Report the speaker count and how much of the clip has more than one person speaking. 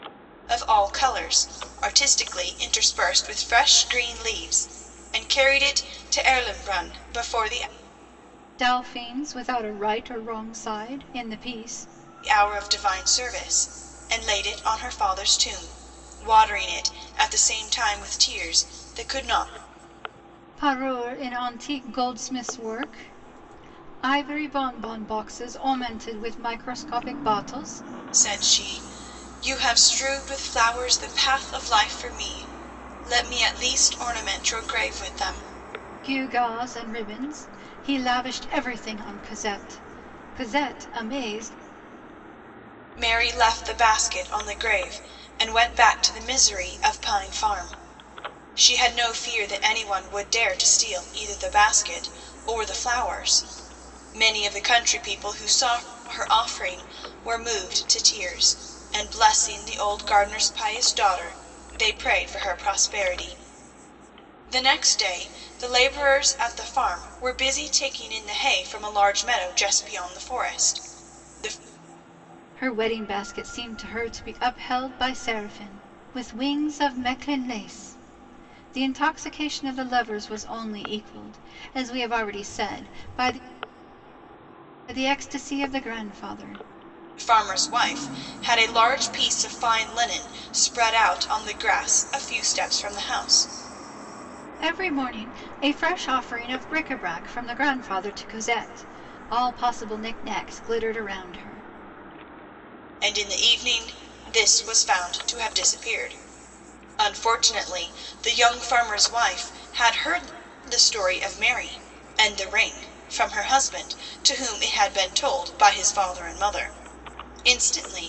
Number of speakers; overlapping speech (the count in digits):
2, no overlap